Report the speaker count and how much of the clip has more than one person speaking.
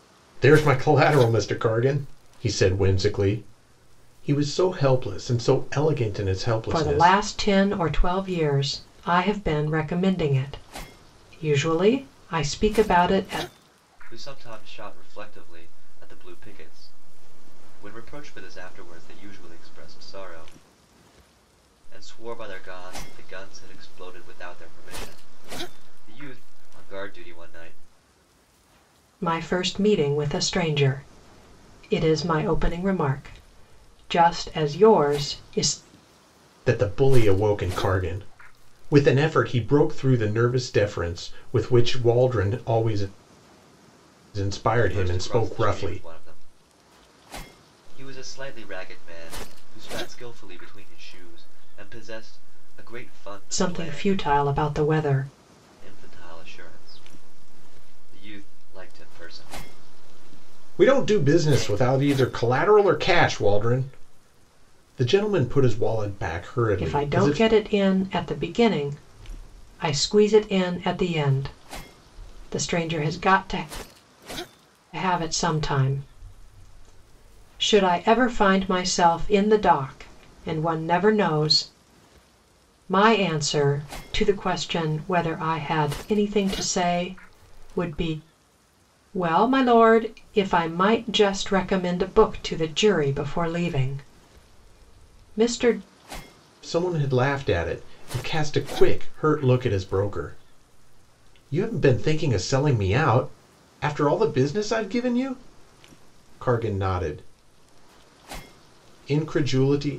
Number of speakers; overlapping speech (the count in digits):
3, about 4%